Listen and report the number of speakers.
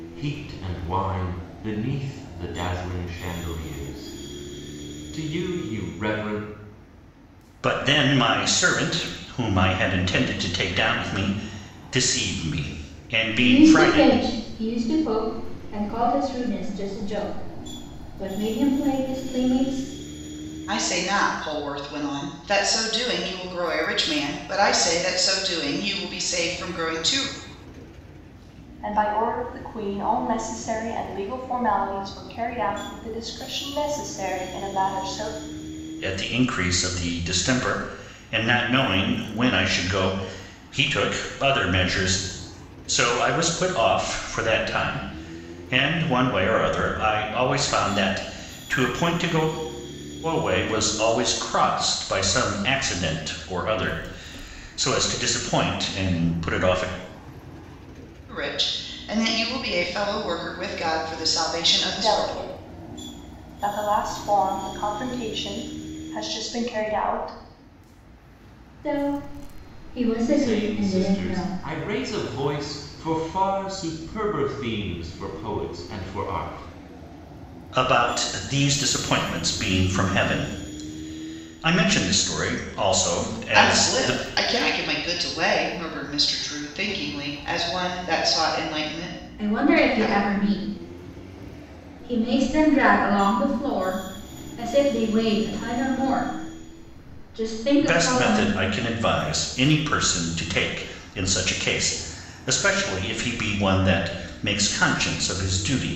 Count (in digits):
5